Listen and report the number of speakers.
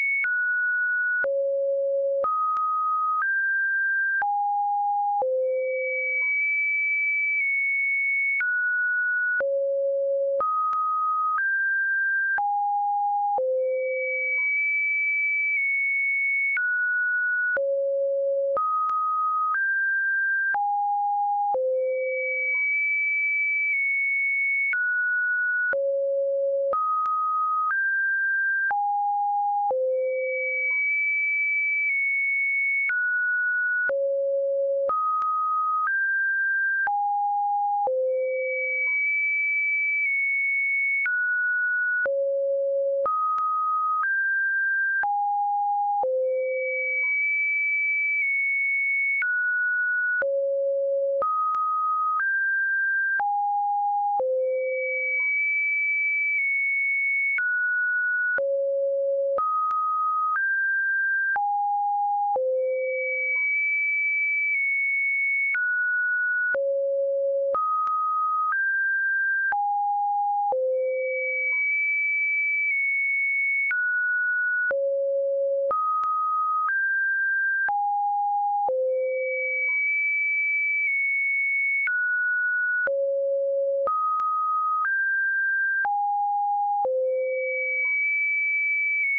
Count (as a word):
zero